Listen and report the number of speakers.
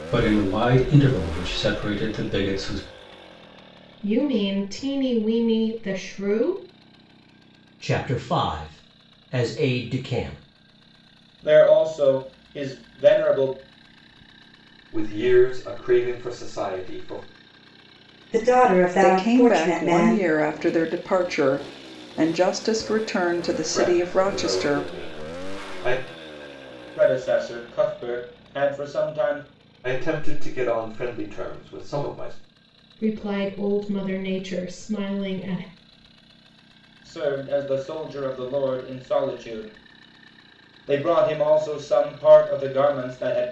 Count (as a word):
seven